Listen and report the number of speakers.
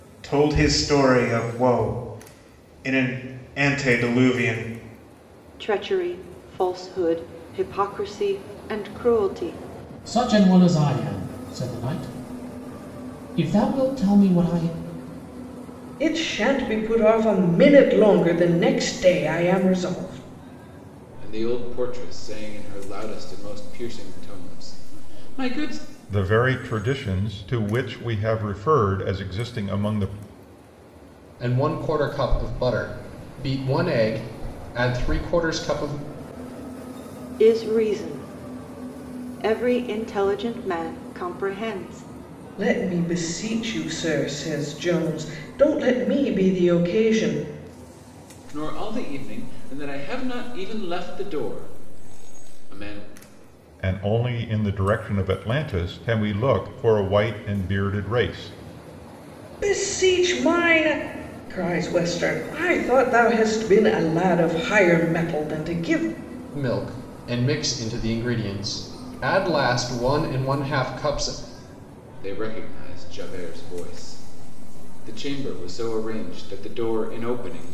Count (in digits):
7